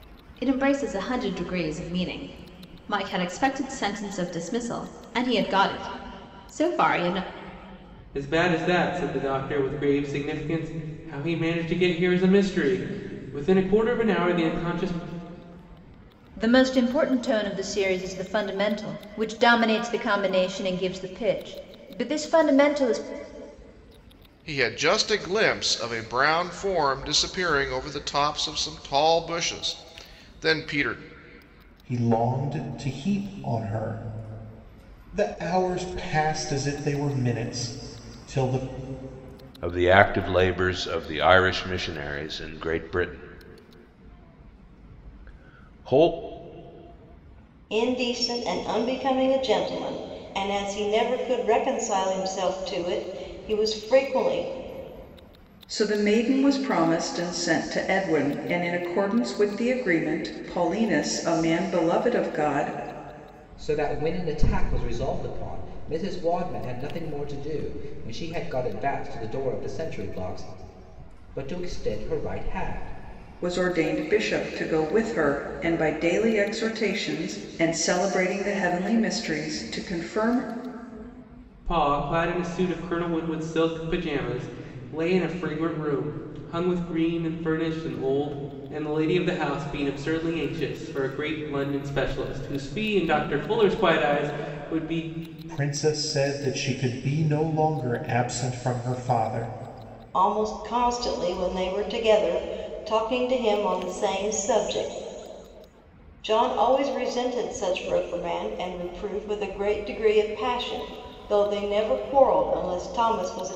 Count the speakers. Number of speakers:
9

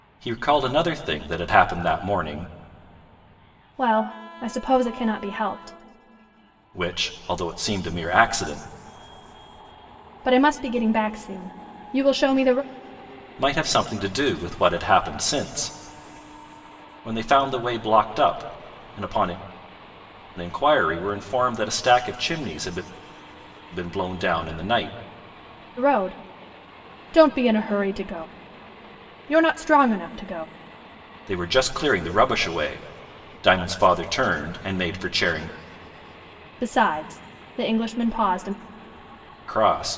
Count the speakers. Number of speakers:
2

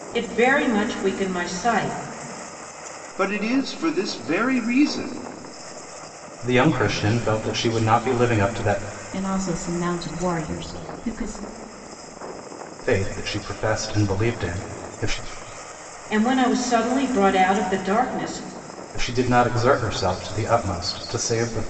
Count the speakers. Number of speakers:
4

